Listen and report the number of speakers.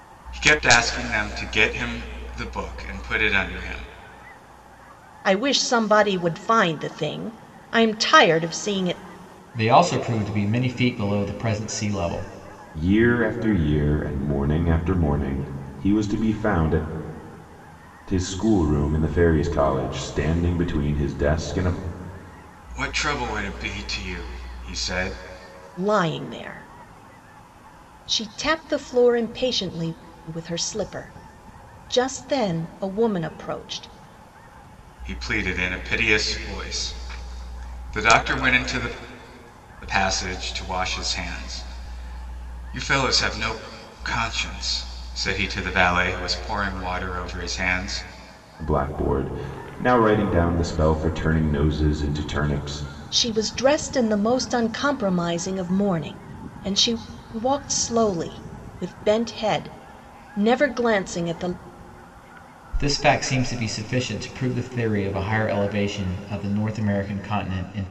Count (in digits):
4